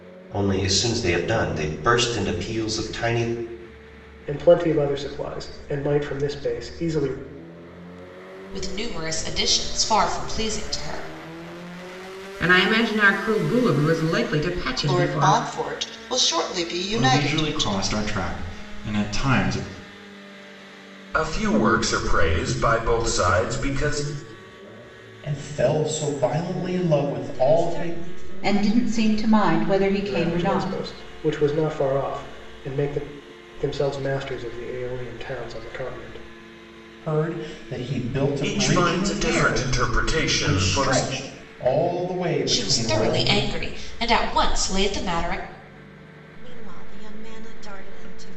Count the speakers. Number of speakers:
10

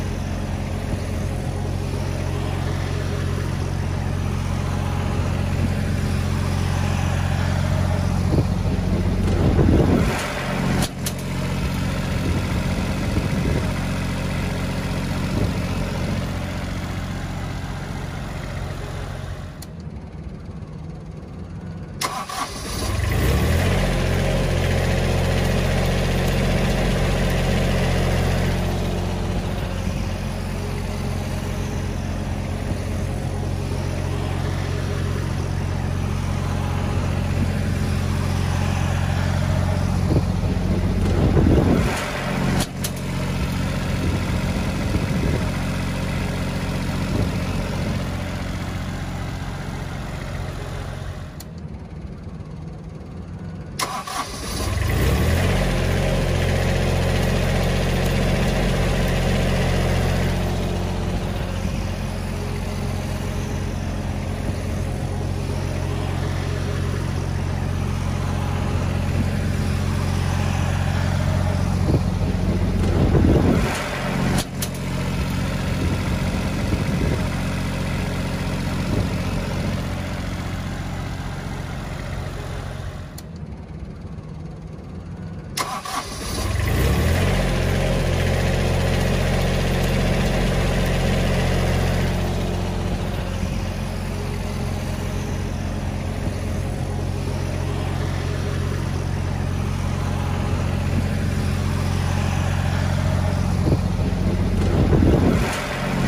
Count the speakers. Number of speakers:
0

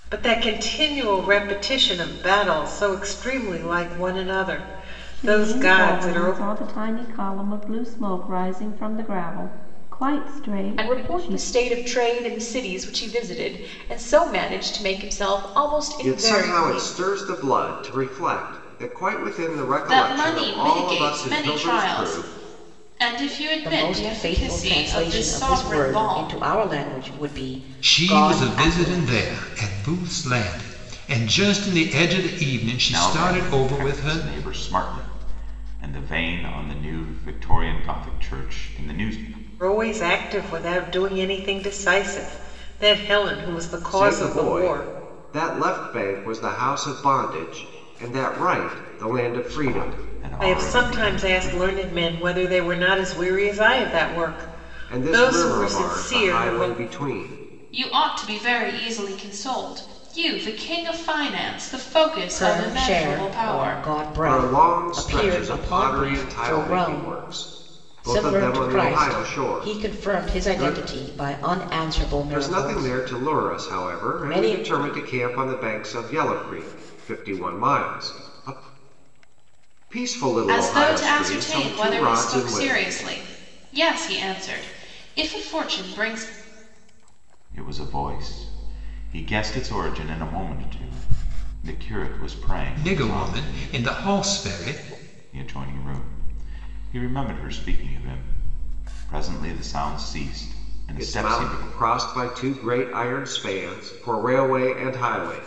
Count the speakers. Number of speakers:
8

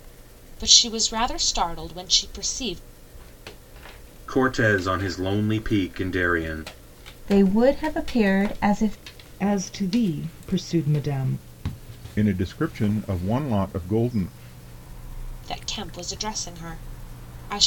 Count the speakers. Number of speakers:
5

